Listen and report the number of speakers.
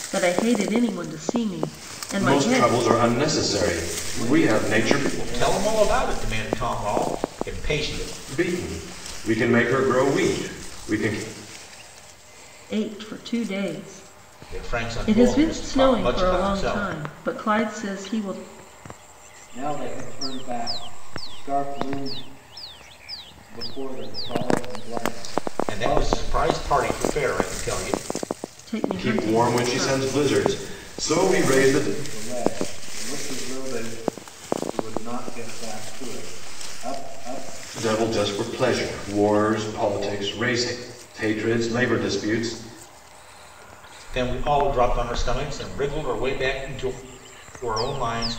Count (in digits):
4